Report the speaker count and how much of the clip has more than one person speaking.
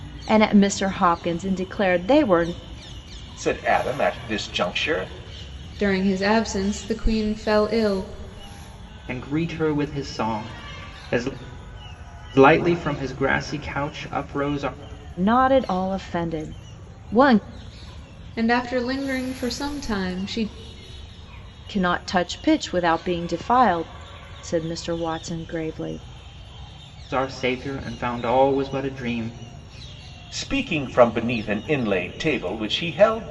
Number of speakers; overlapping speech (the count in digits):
4, no overlap